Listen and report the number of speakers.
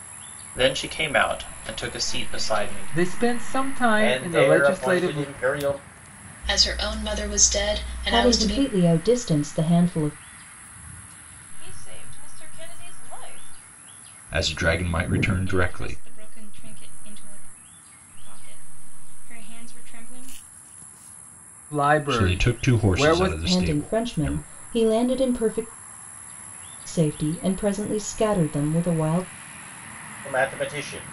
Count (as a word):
eight